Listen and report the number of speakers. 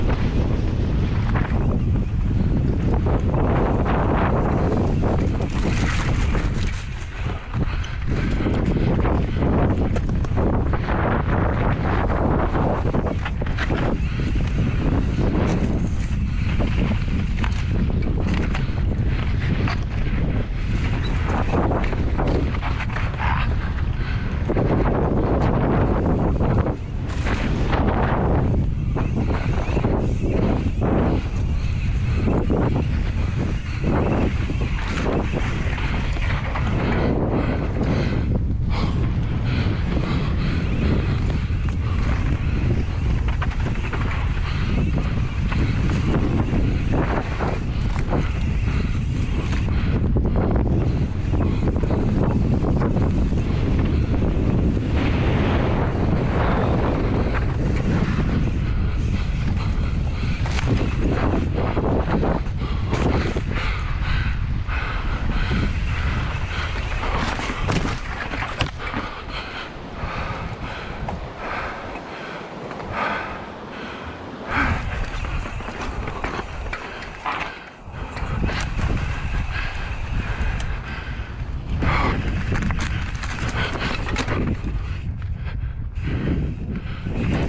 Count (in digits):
0